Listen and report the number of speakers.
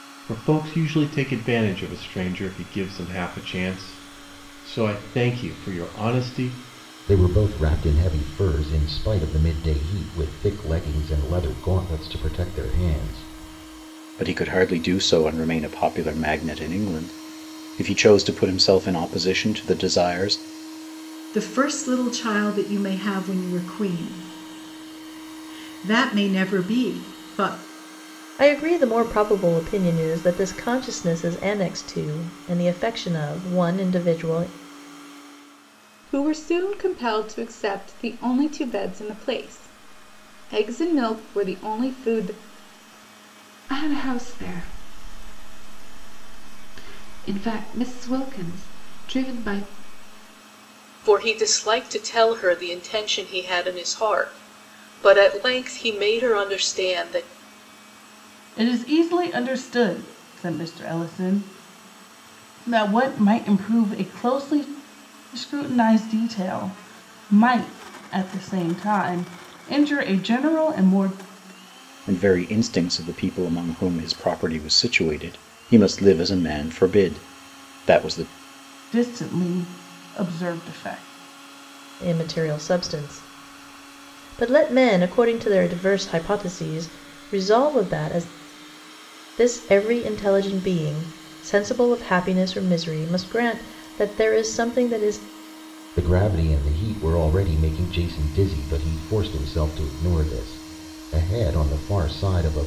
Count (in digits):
9